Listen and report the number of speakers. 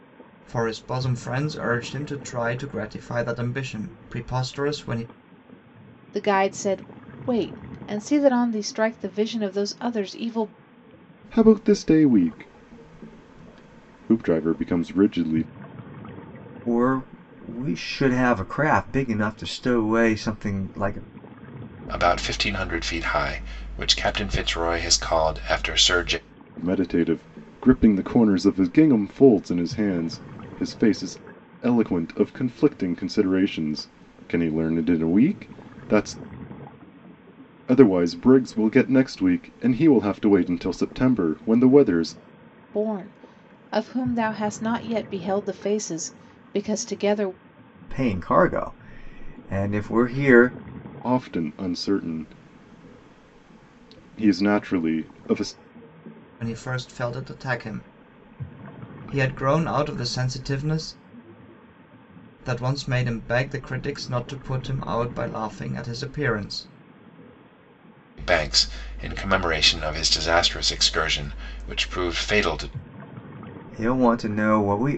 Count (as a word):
five